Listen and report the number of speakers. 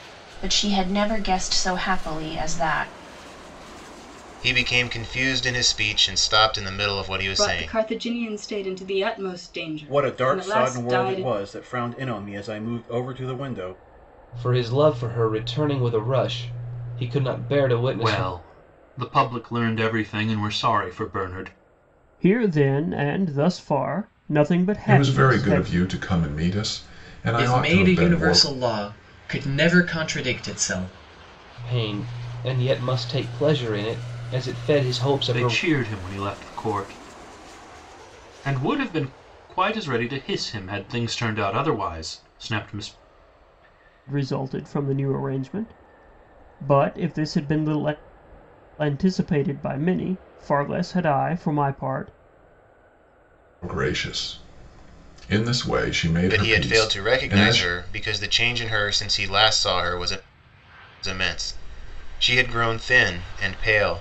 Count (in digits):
9